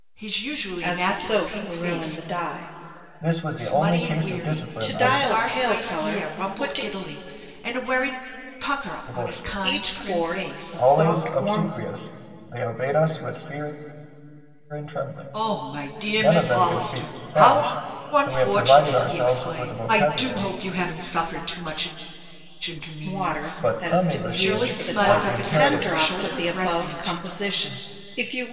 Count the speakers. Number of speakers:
3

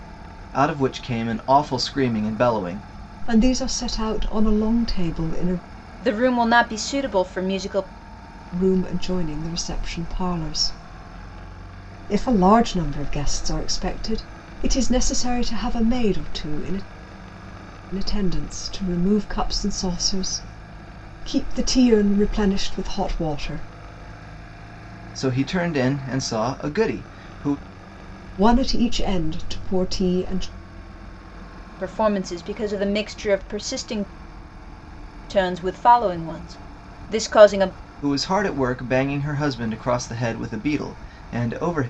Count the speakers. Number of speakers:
3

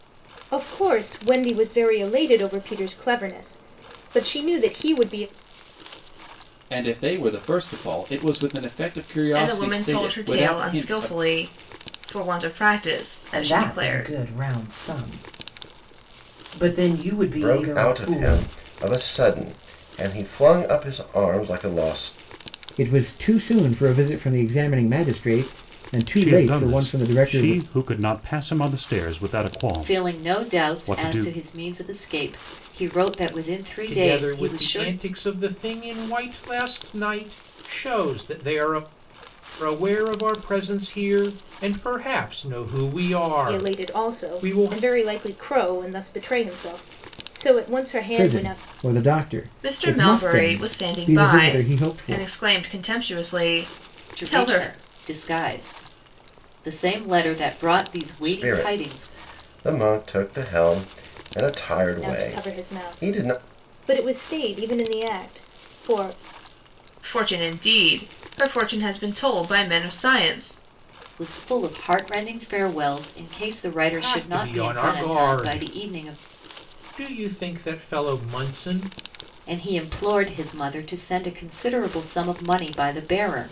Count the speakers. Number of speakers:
9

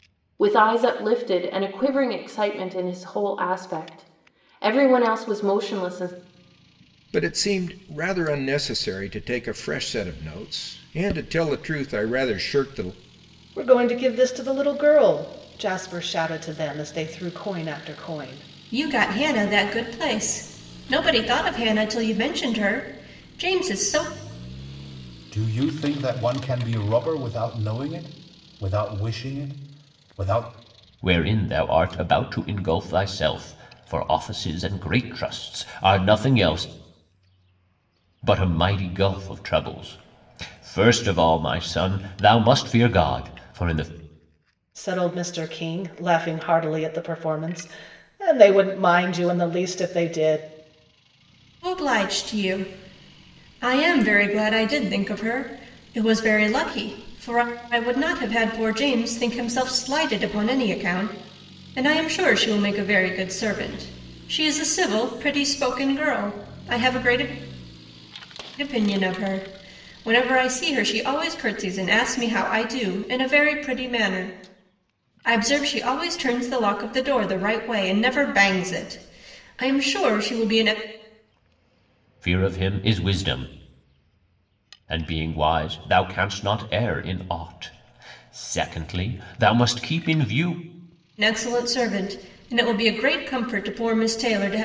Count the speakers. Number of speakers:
6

